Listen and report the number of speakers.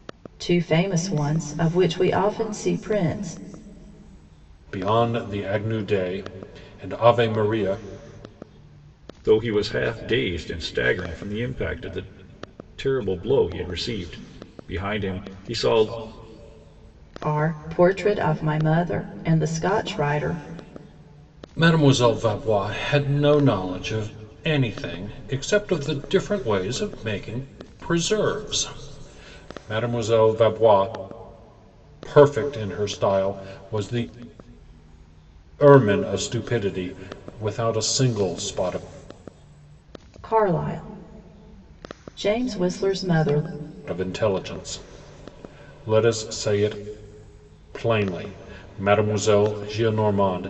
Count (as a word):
three